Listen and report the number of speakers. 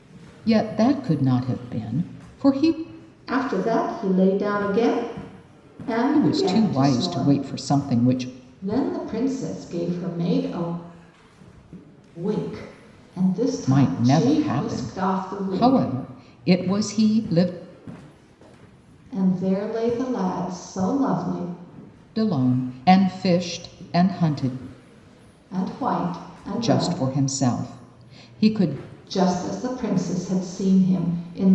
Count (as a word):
two